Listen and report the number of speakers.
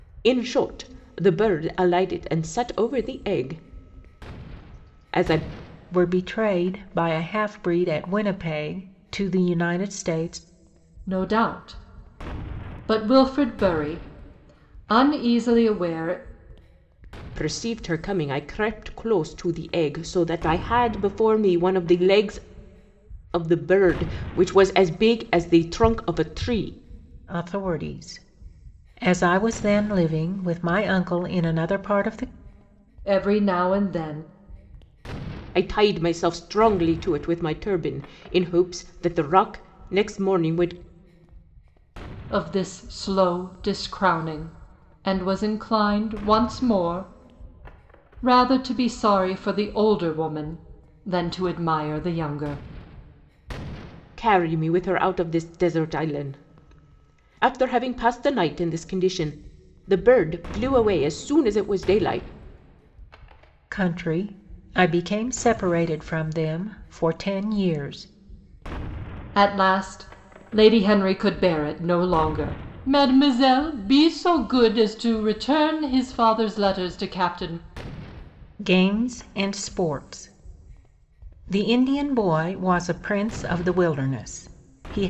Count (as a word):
three